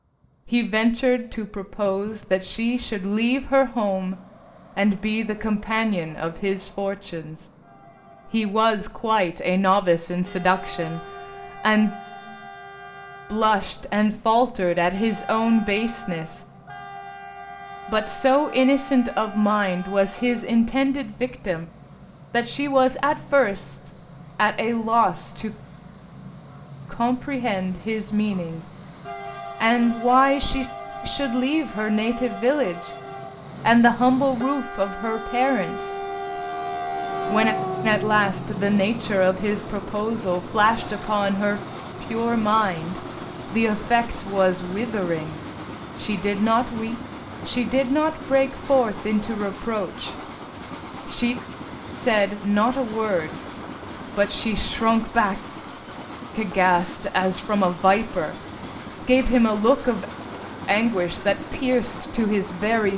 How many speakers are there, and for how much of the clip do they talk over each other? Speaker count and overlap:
one, no overlap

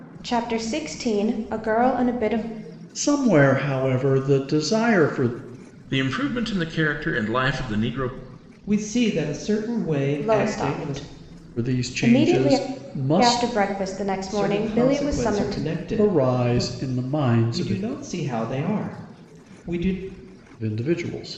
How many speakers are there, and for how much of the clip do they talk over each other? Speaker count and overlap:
four, about 22%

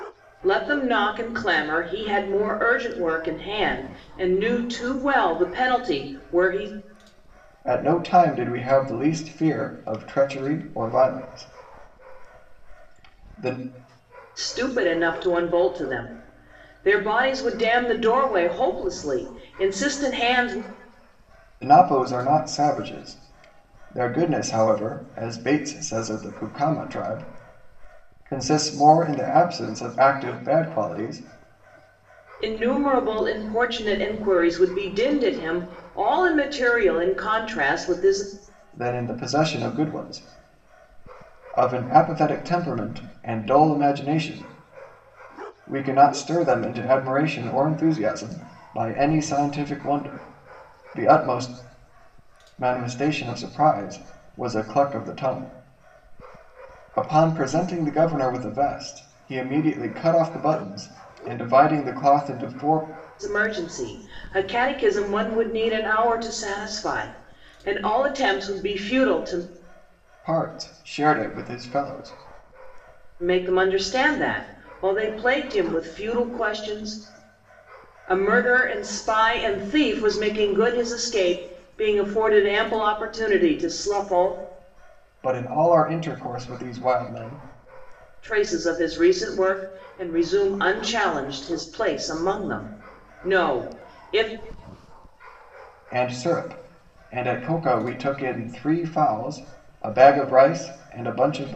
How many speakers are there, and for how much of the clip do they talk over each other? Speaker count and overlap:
two, no overlap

